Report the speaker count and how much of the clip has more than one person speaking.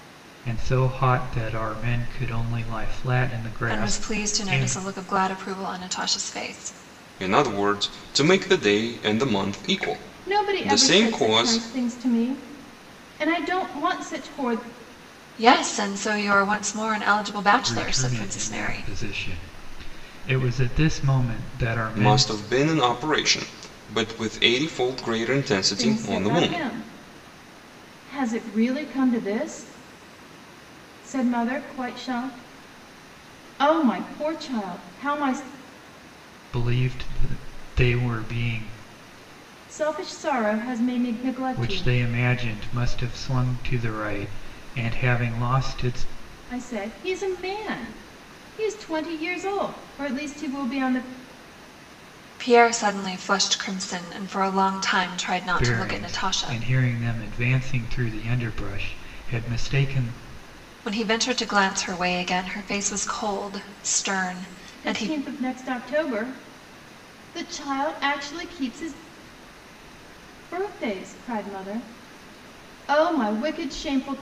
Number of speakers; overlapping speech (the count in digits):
4, about 9%